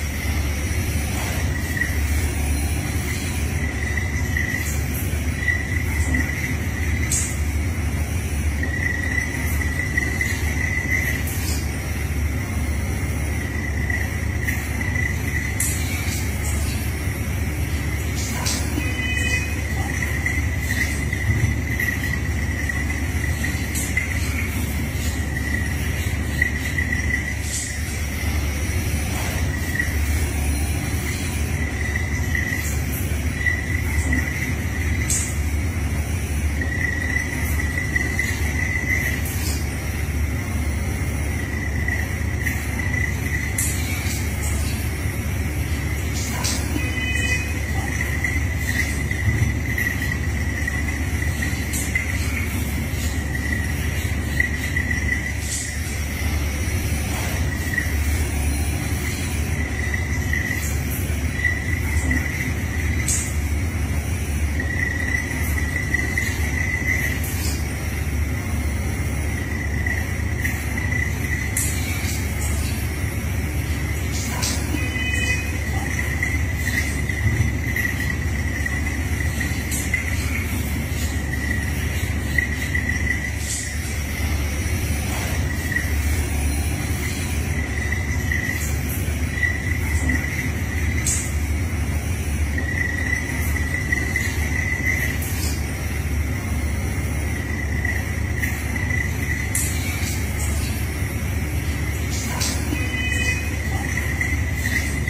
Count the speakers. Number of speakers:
0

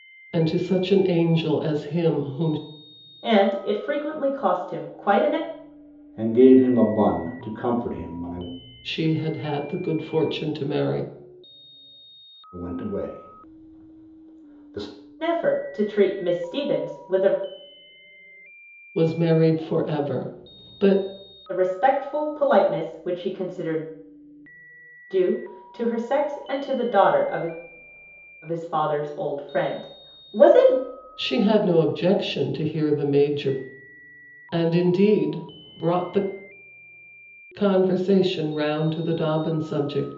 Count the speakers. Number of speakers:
3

